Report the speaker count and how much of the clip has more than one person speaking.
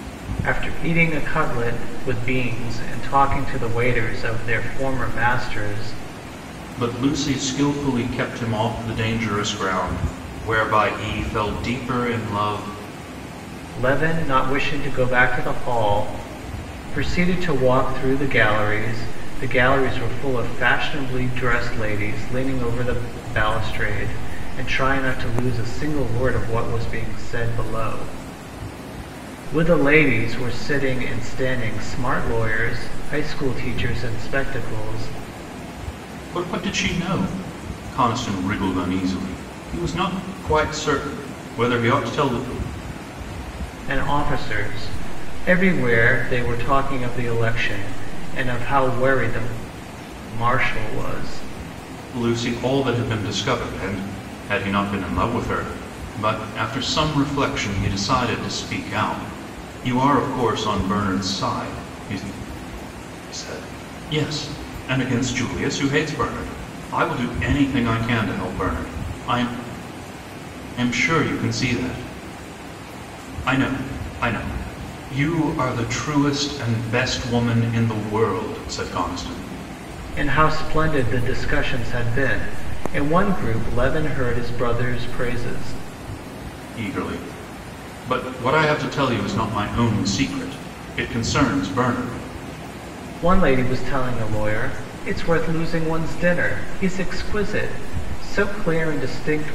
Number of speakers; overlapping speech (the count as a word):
two, no overlap